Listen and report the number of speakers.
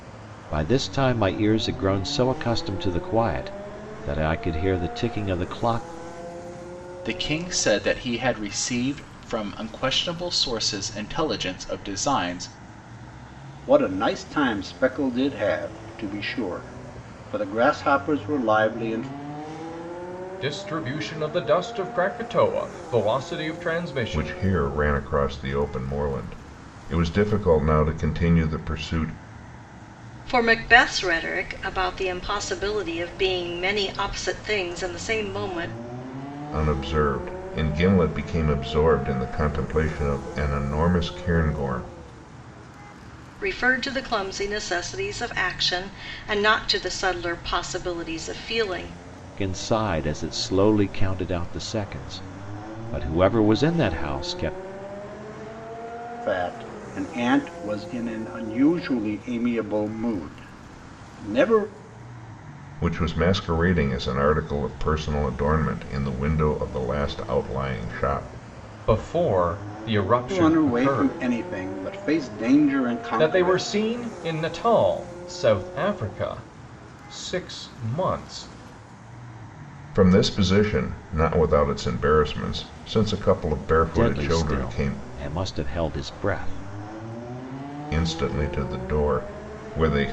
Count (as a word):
six